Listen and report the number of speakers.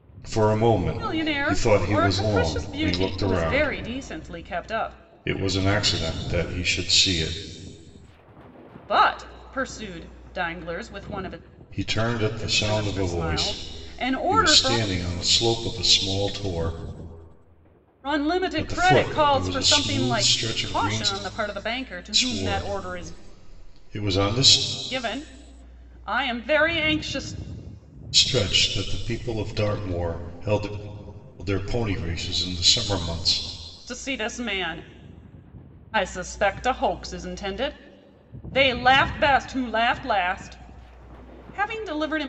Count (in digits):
2